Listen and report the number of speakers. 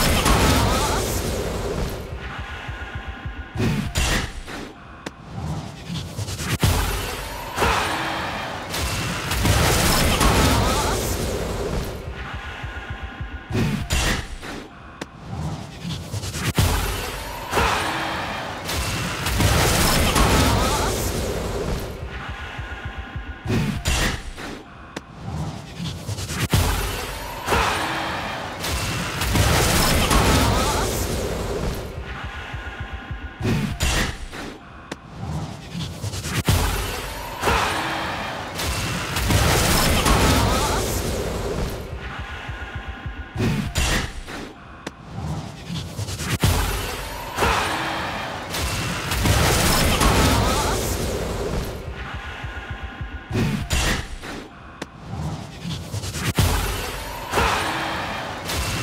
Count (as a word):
zero